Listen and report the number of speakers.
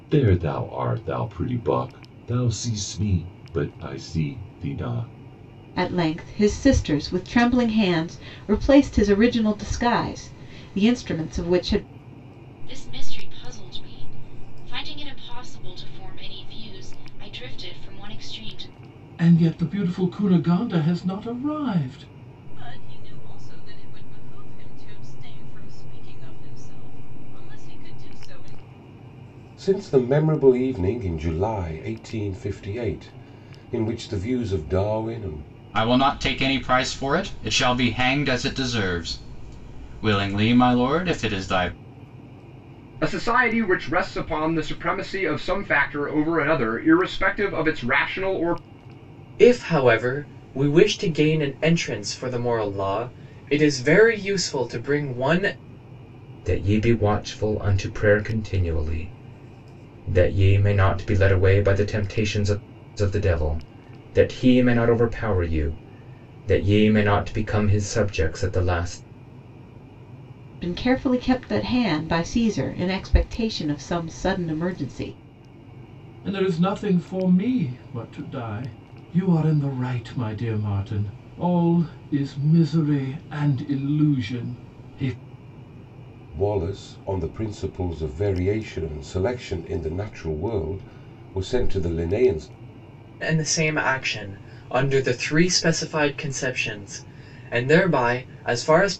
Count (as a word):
ten